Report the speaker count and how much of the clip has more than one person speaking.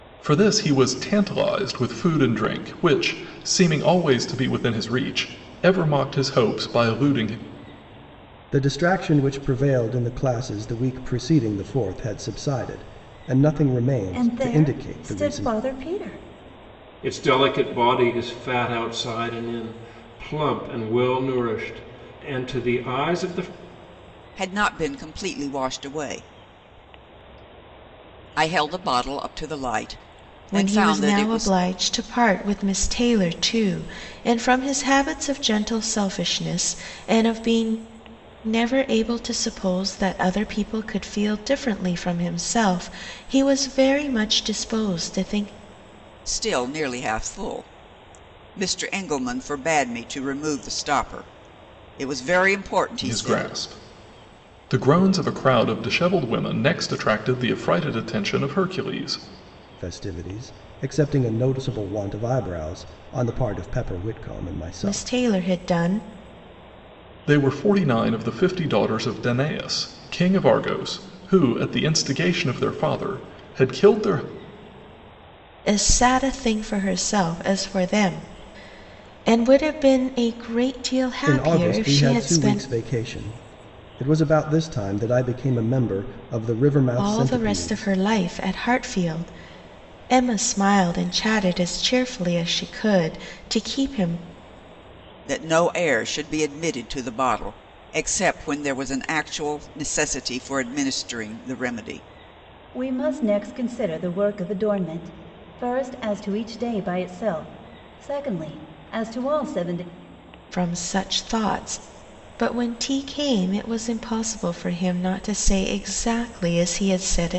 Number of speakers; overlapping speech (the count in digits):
6, about 5%